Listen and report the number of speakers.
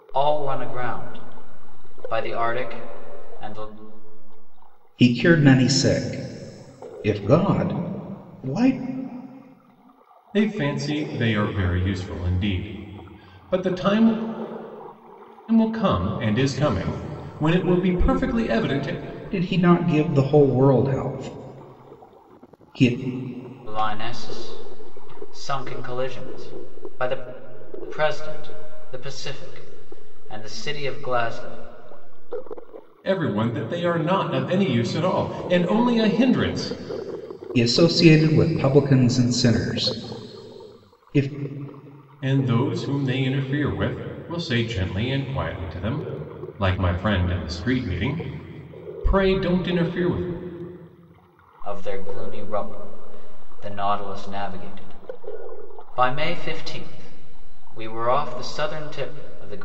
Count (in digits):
3